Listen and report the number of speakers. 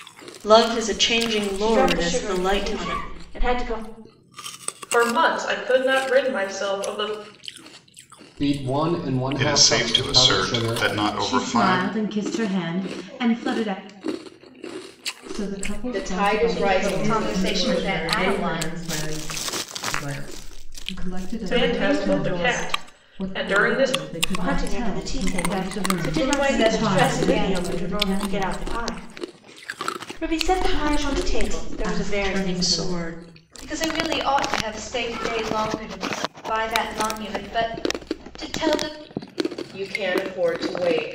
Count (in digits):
10